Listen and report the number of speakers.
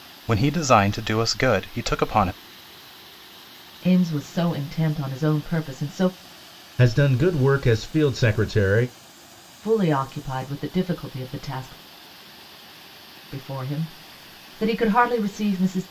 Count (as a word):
three